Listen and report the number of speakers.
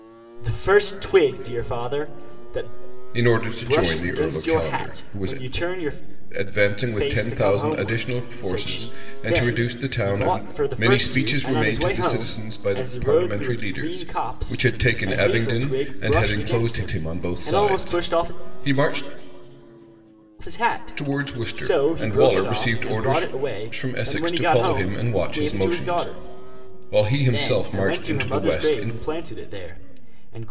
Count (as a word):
two